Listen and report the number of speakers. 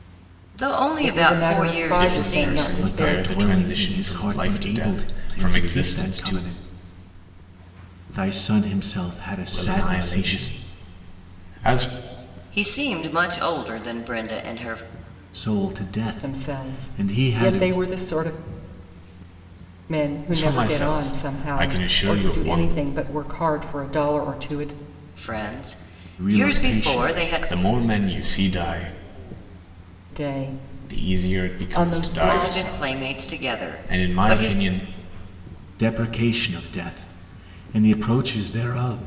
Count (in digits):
4